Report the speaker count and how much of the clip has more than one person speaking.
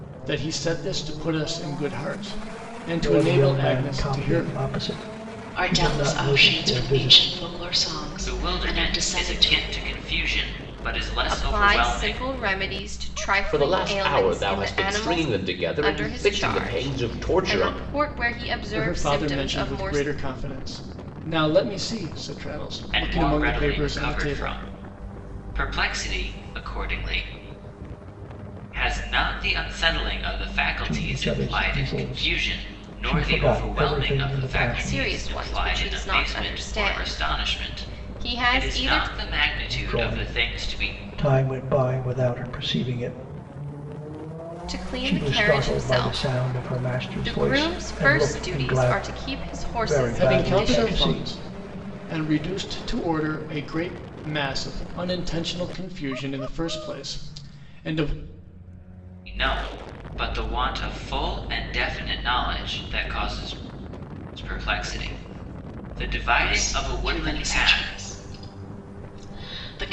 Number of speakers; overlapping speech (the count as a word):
six, about 40%